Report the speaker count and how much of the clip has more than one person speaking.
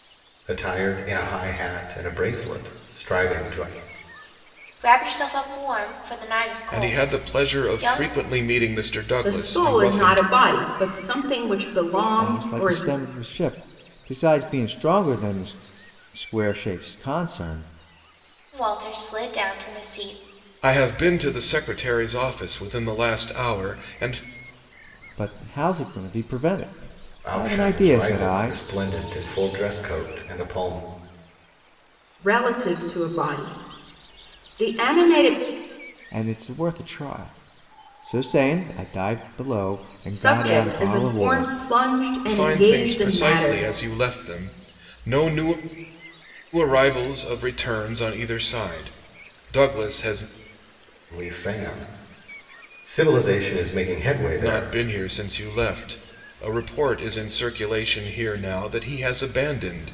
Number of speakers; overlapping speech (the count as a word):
five, about 13%